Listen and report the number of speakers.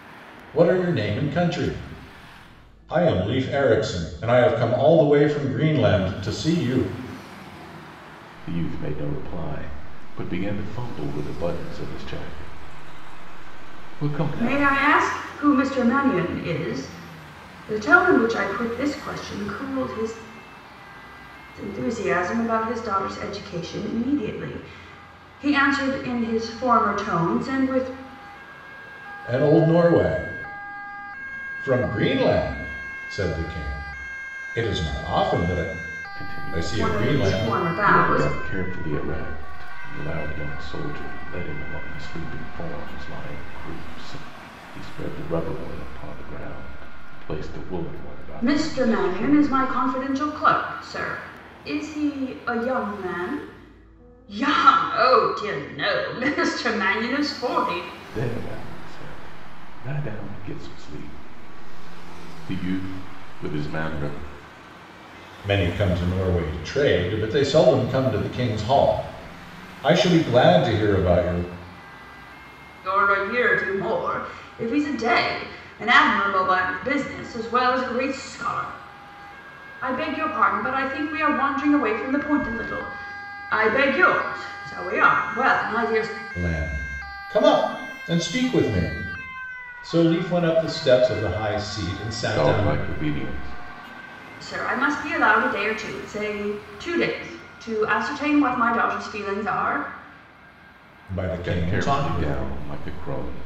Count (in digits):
3